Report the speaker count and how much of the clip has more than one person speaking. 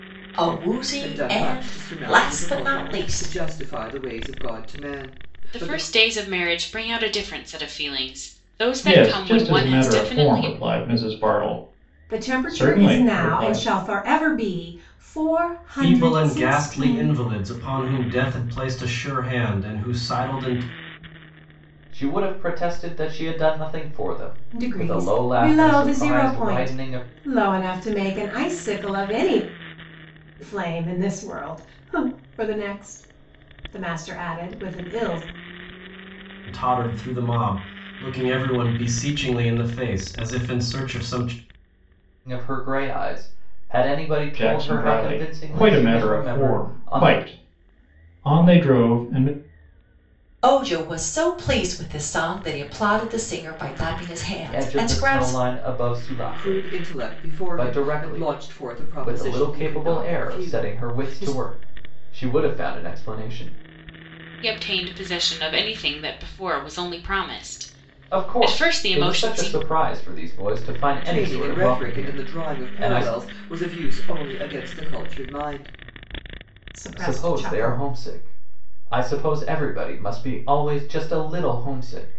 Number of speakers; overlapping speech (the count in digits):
7, about 28%